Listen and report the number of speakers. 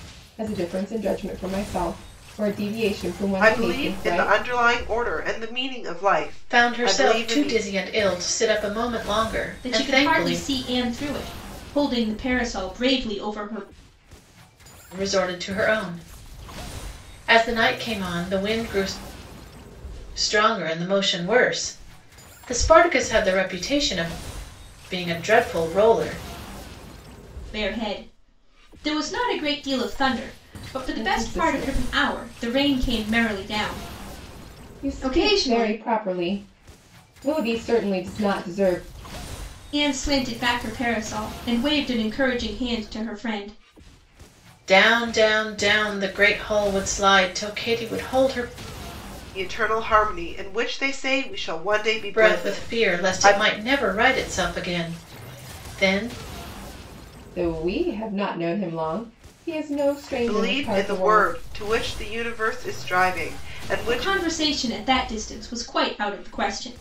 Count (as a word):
four